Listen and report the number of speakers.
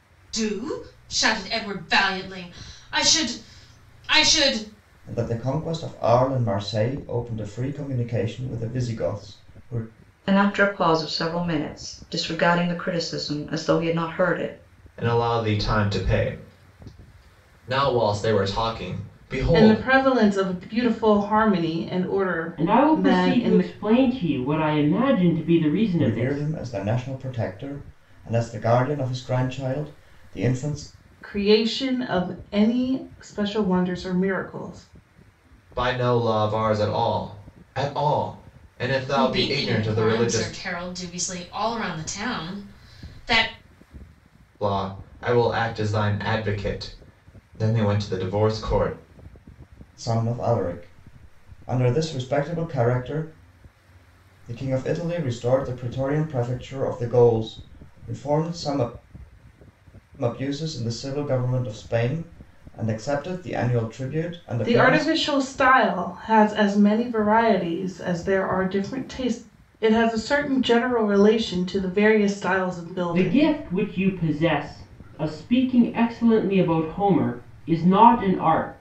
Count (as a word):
six